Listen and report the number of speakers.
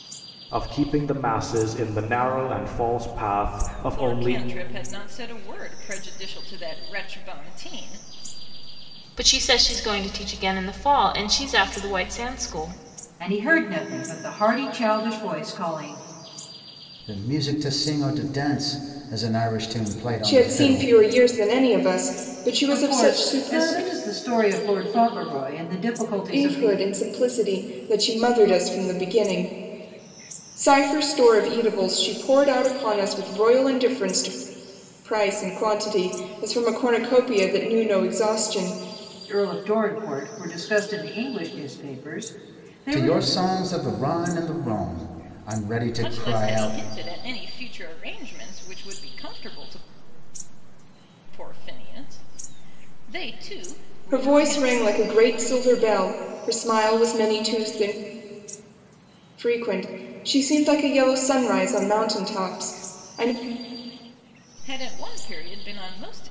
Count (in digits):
6